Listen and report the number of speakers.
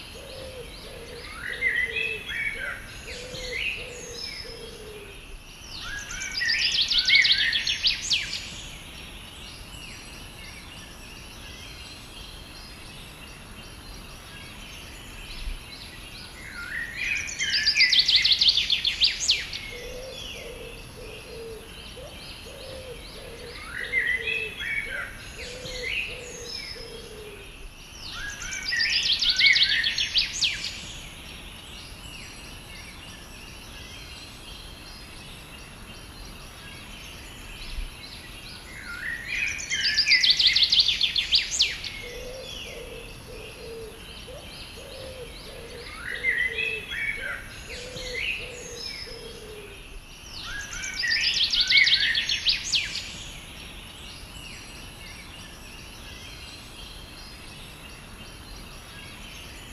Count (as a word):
zero